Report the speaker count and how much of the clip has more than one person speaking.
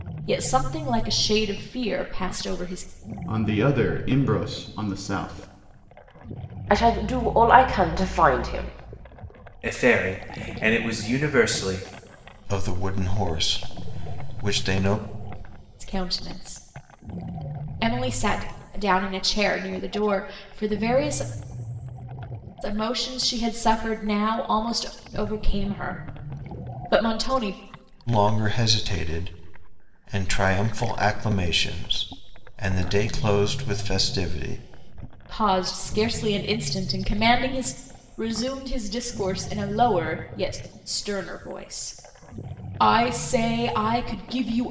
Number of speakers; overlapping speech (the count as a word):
five, no overlap